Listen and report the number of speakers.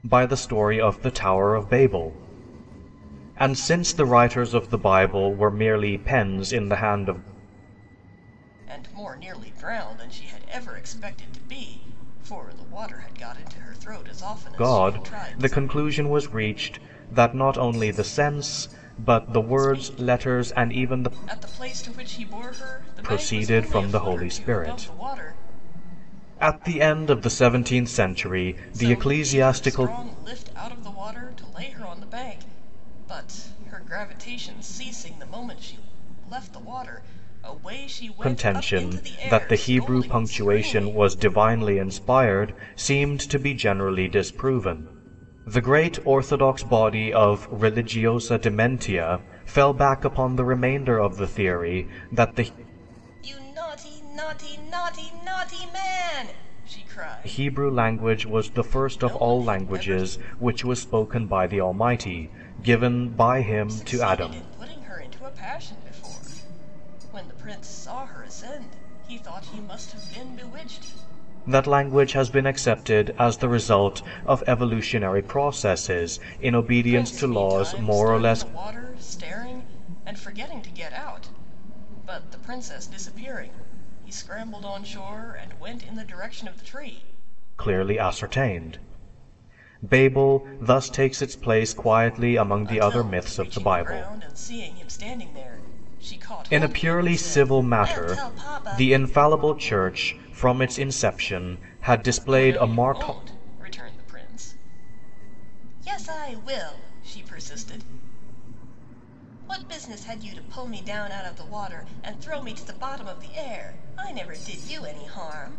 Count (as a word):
two